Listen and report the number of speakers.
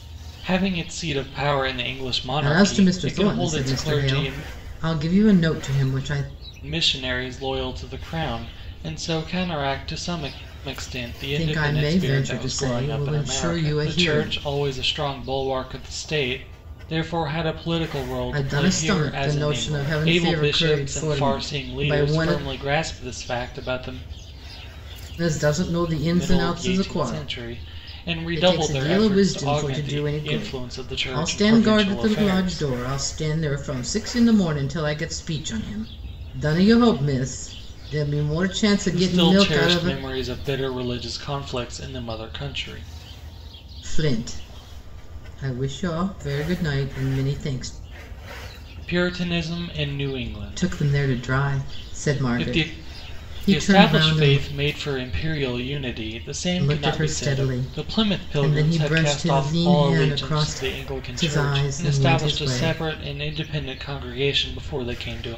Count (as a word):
two